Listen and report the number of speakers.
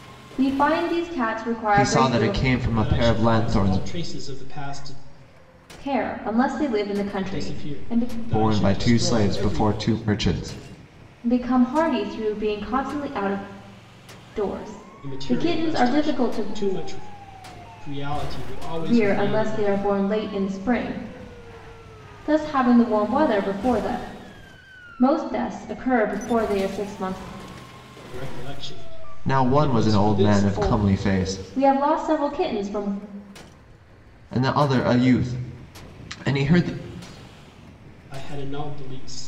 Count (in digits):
3